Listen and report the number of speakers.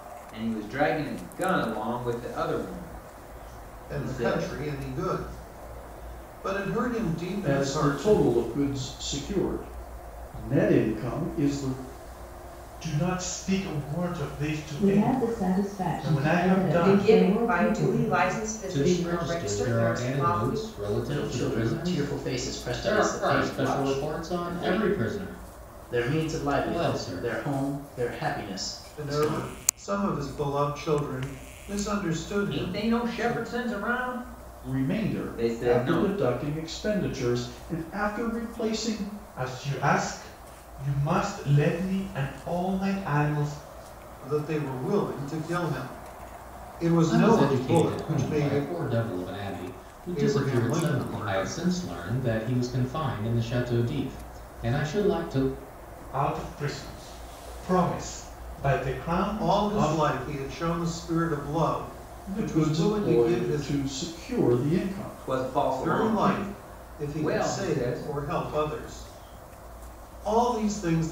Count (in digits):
8